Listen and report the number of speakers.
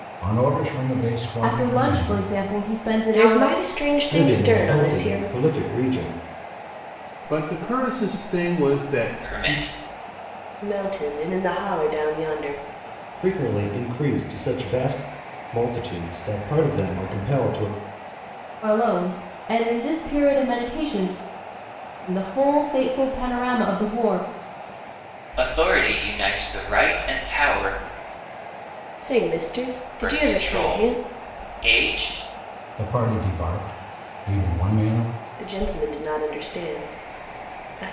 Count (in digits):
6